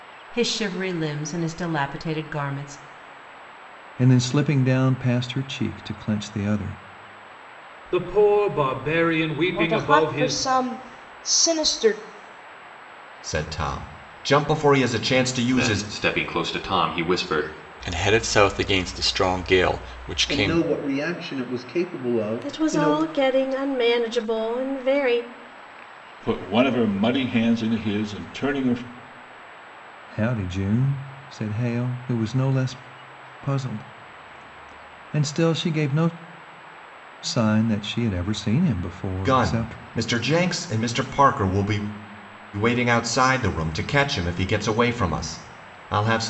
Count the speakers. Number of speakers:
10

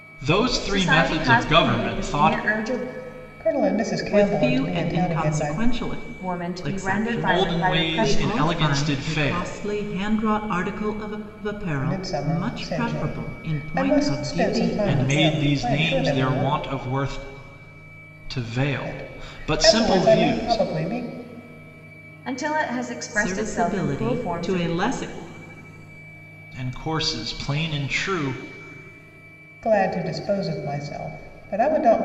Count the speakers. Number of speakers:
4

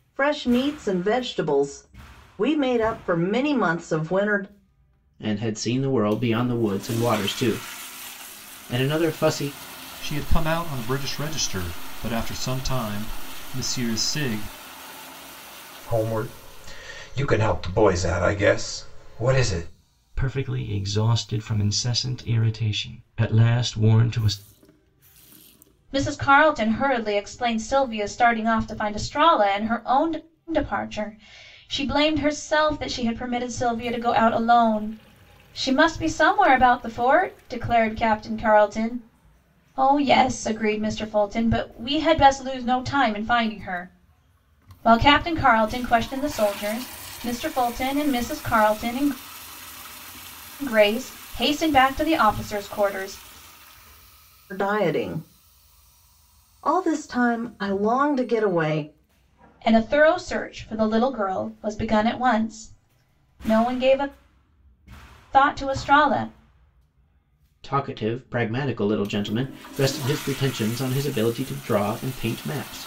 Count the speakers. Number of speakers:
6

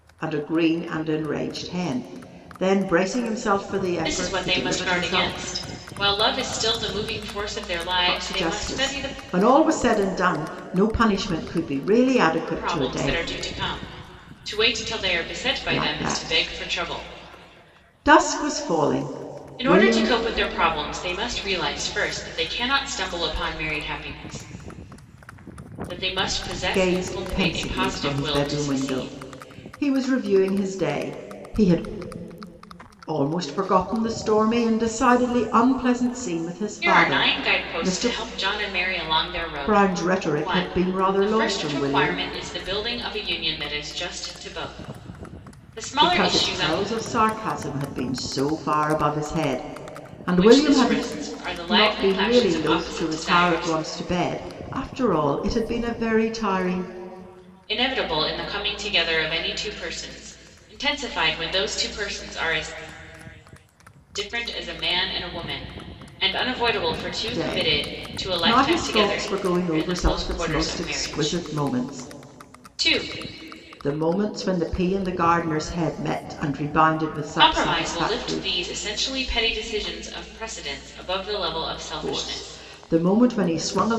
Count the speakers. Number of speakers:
2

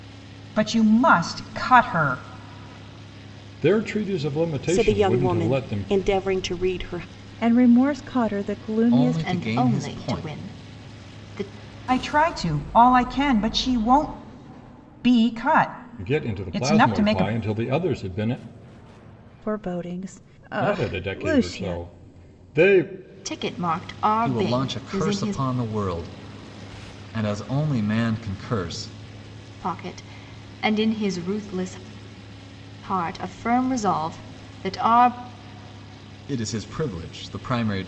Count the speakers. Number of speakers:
6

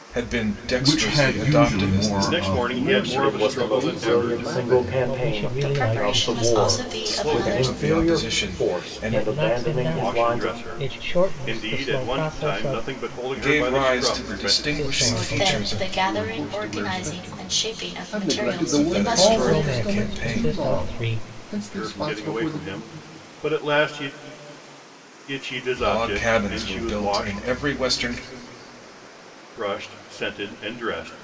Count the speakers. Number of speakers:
7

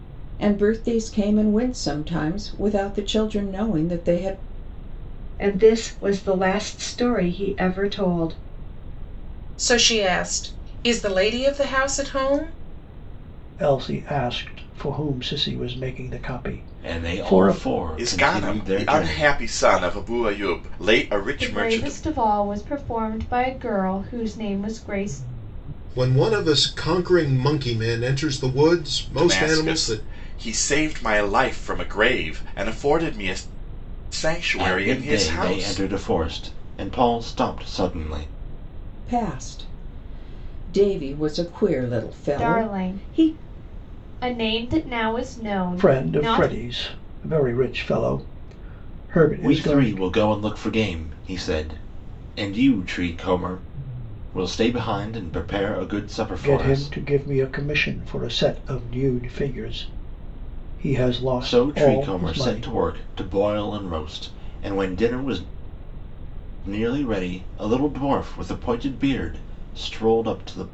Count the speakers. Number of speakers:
8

